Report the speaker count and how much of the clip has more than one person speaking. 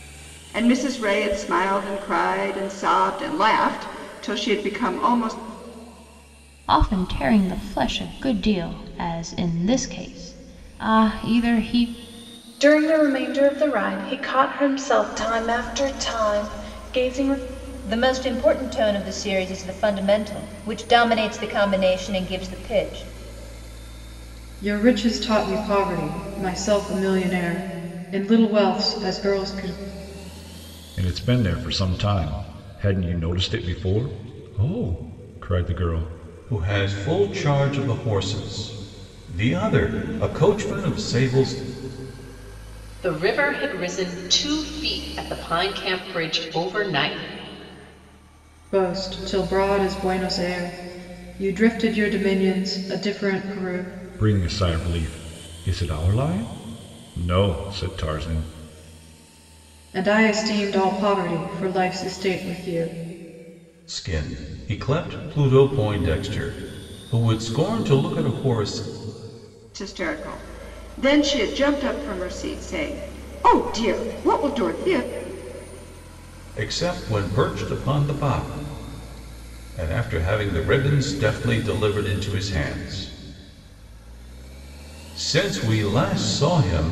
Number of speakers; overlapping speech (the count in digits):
8, no overlap